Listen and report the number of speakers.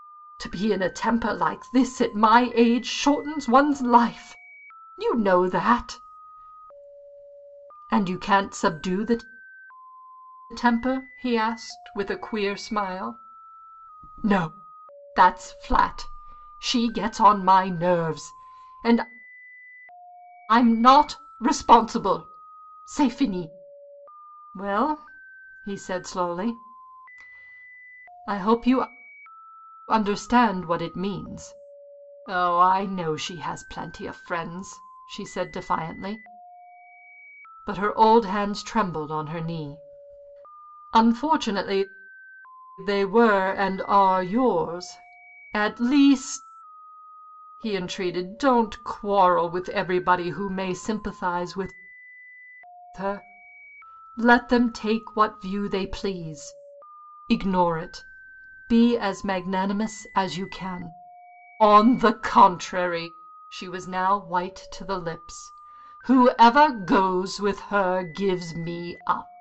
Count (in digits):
1